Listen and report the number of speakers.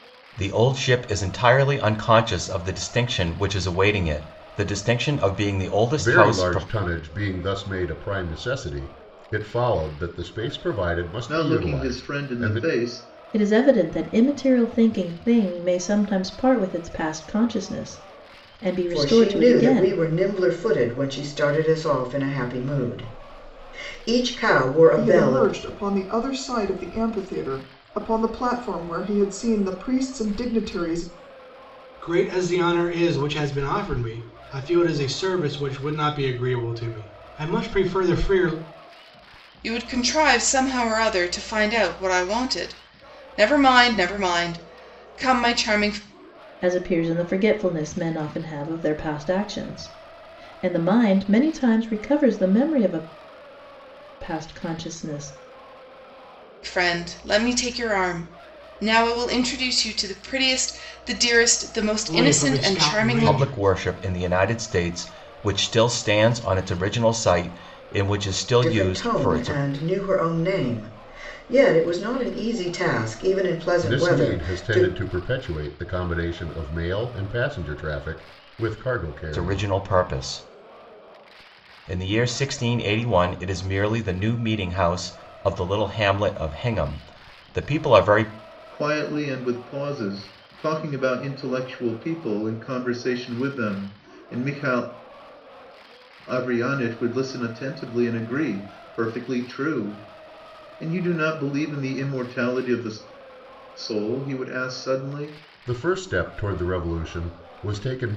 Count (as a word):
eight